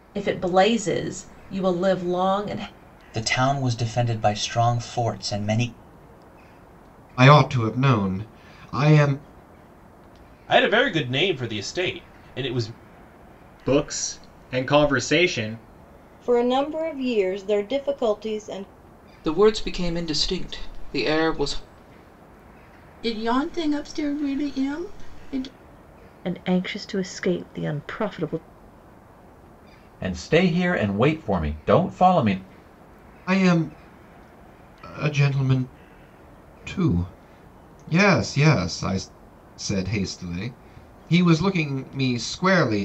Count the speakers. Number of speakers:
10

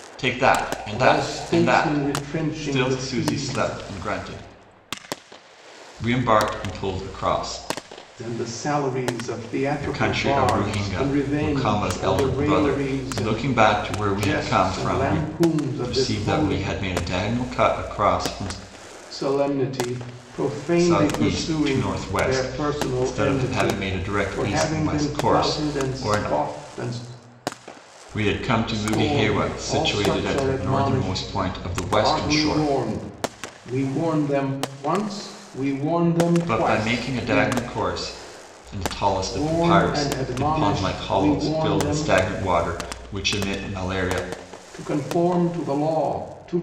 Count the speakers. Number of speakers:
2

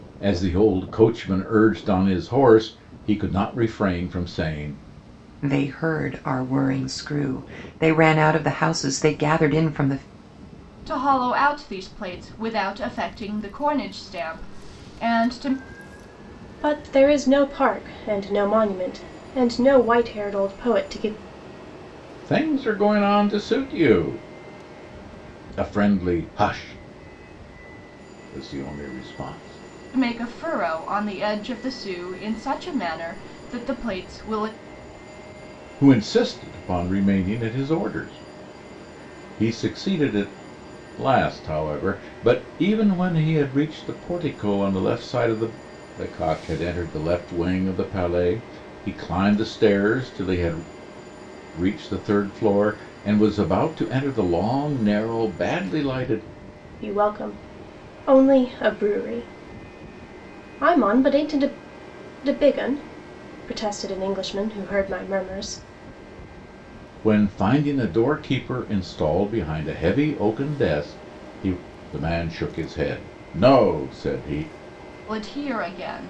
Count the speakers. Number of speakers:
4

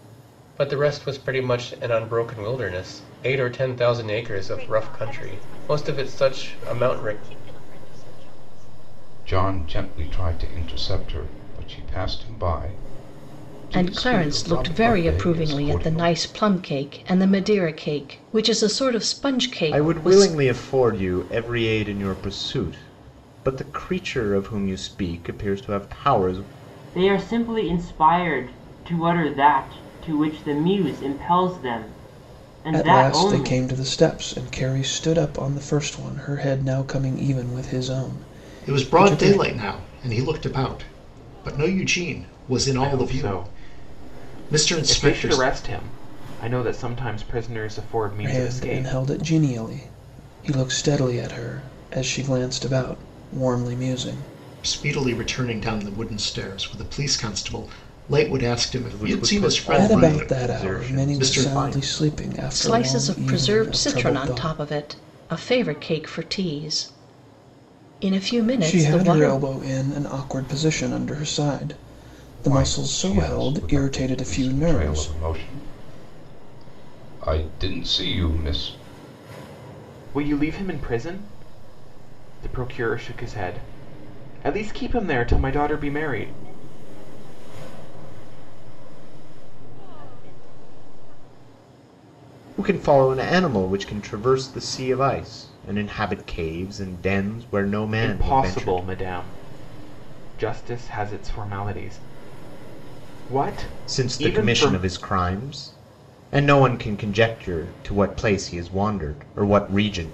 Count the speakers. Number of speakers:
9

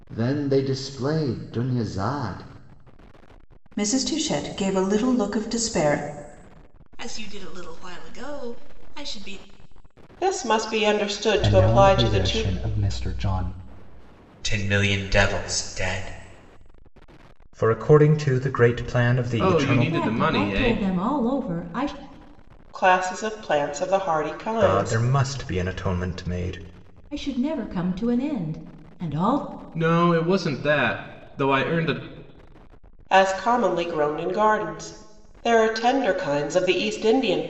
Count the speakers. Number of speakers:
9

